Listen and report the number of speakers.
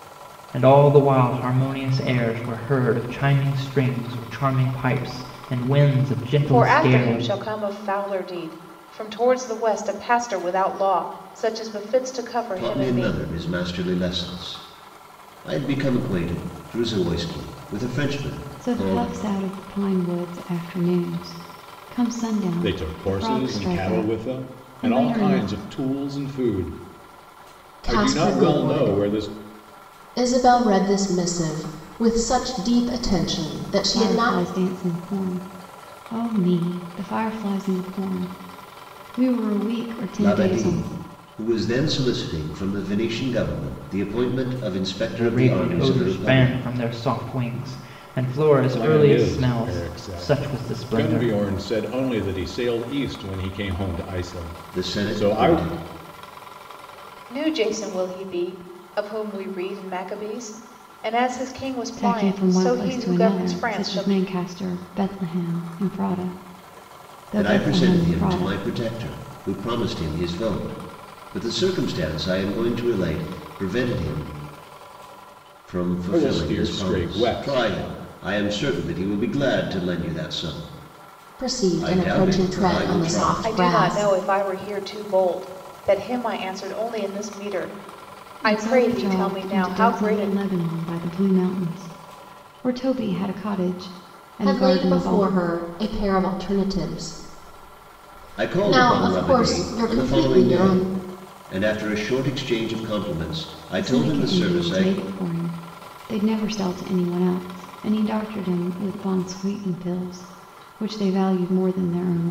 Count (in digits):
6